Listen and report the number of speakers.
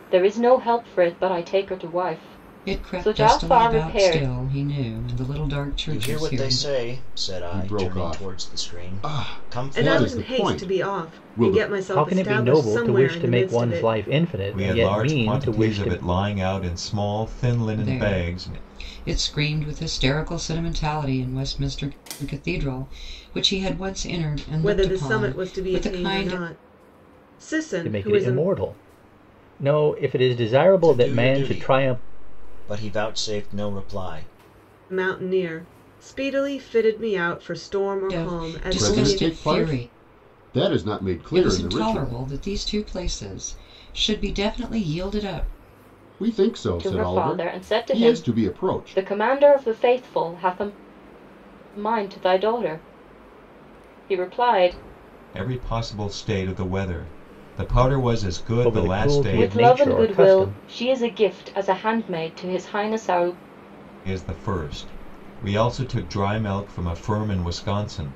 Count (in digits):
7